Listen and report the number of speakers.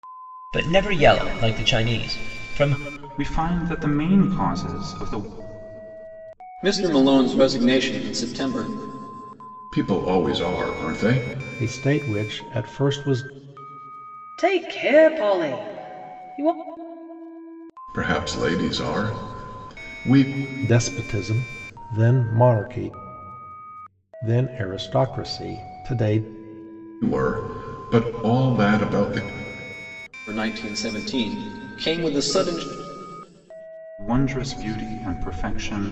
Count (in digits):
6